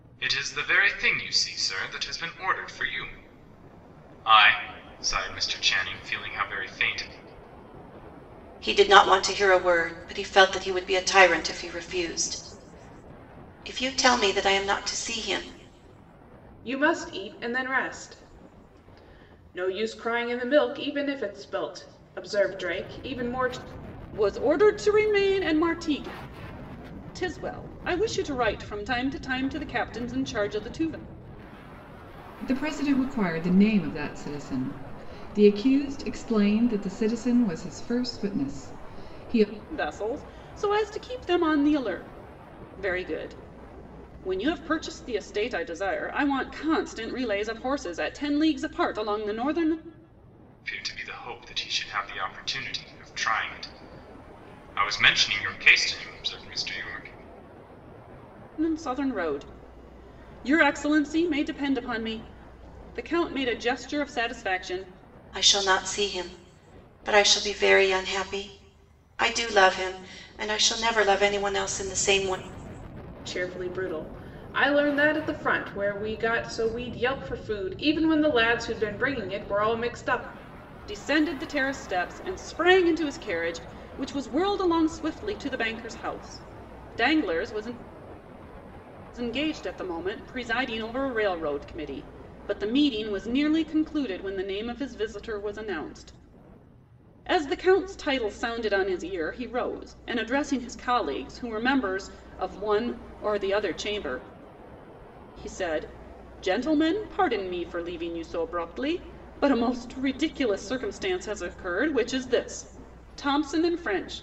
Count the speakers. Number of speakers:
5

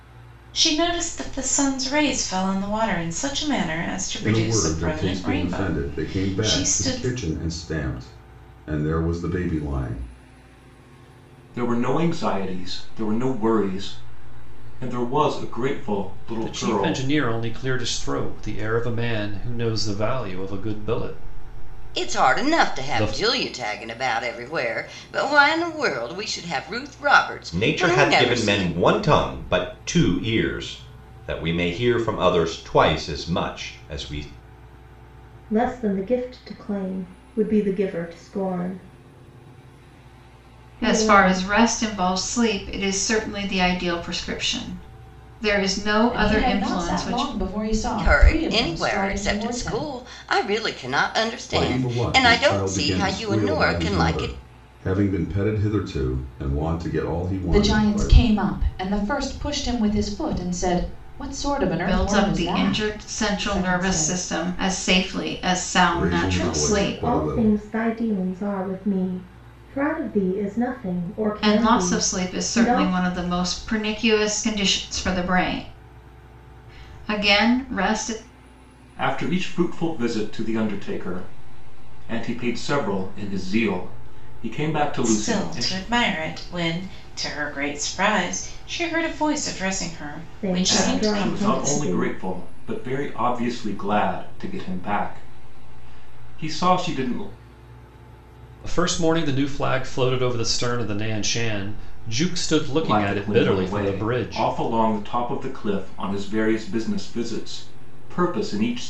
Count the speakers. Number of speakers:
9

